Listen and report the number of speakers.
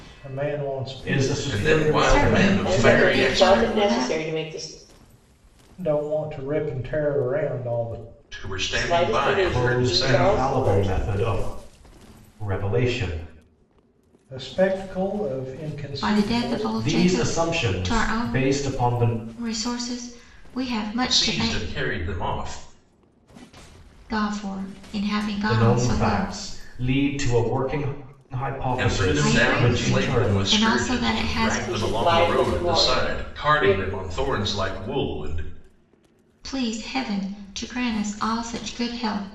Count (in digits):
5